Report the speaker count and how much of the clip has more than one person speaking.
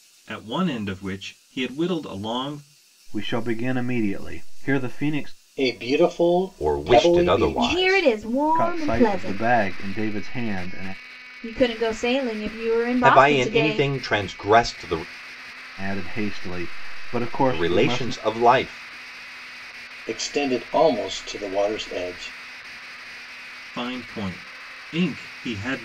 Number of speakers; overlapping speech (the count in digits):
5, about 16%